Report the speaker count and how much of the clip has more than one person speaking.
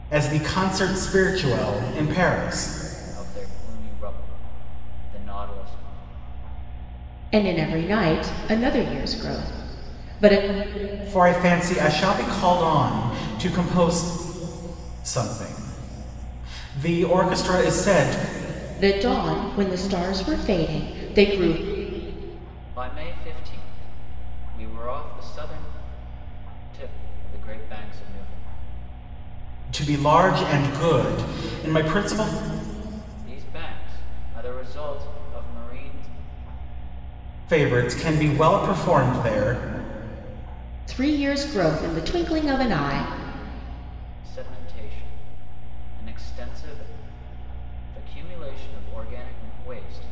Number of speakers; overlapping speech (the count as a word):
three, no overlap